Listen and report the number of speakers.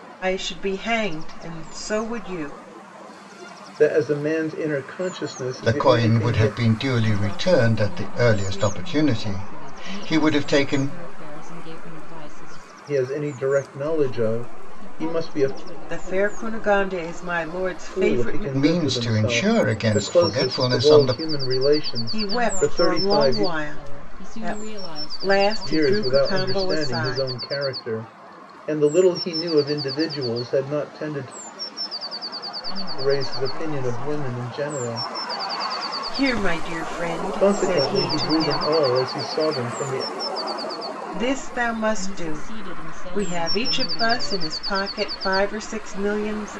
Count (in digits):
4